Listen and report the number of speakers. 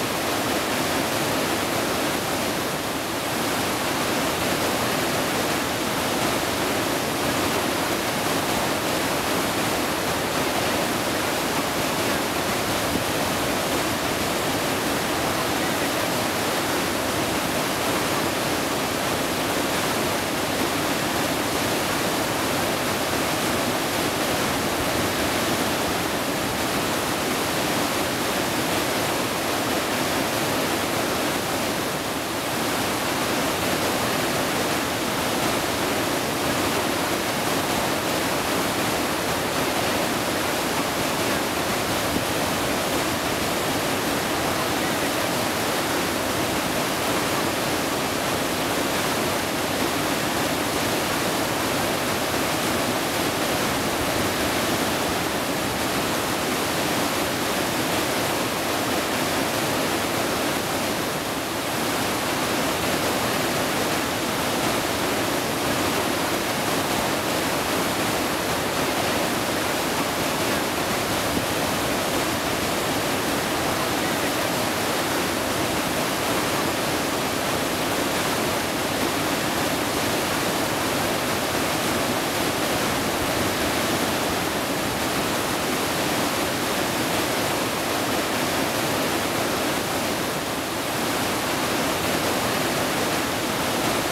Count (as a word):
zero